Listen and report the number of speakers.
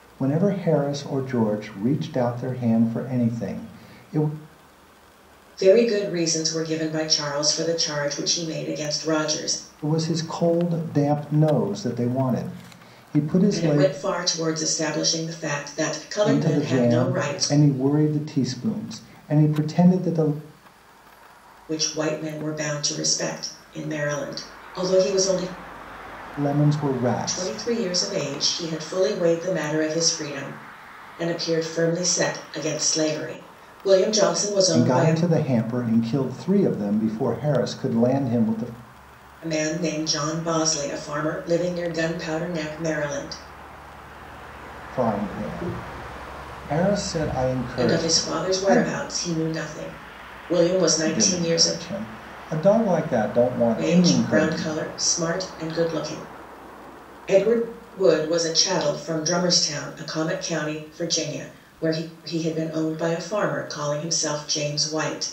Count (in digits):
2